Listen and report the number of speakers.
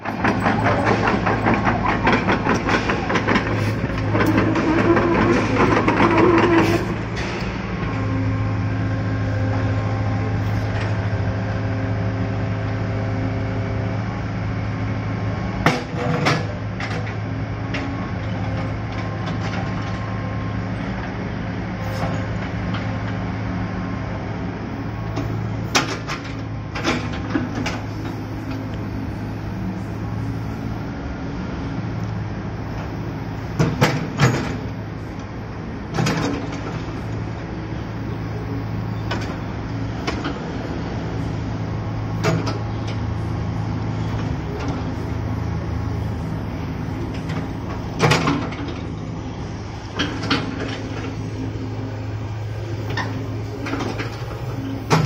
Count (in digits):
0